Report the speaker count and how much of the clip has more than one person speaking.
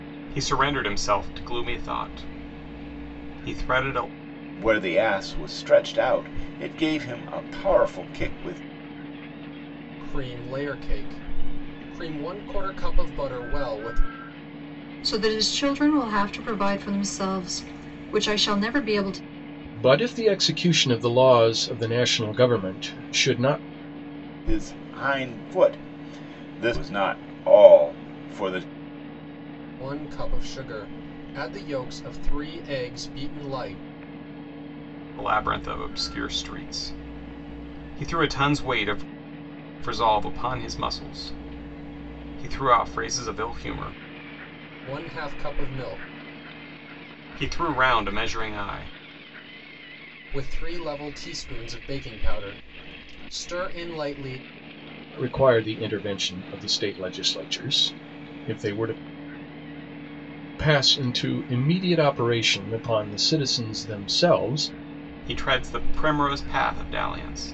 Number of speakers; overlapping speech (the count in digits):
5, no overlap